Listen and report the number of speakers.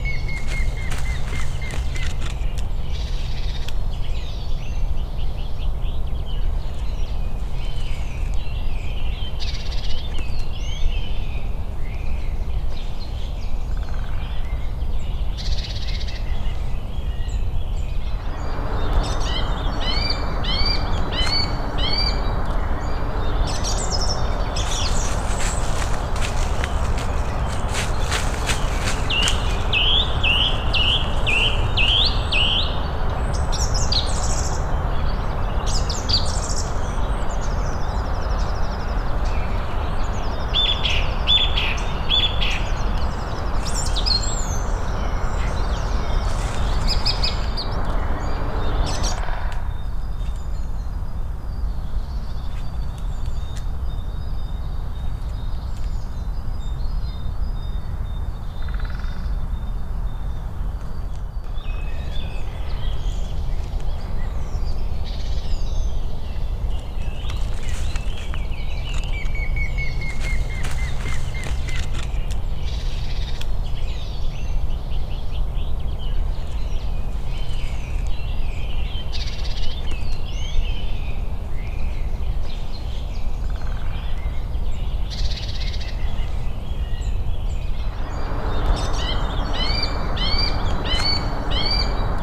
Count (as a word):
zero